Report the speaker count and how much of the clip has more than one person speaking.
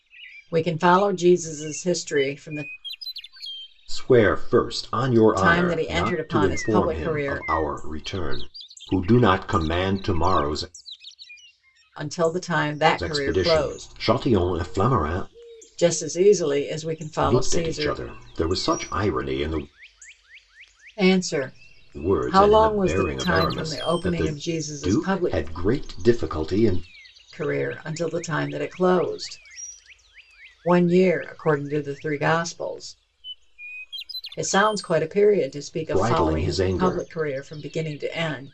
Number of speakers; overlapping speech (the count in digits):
2, about 21%